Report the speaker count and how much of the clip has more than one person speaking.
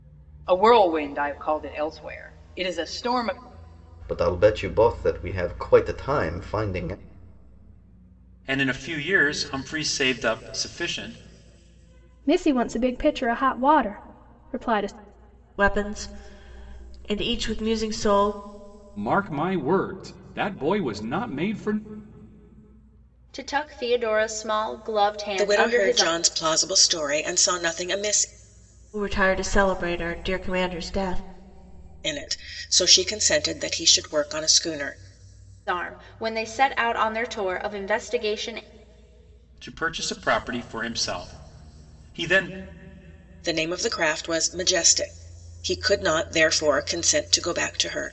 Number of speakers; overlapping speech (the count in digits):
8, about 2%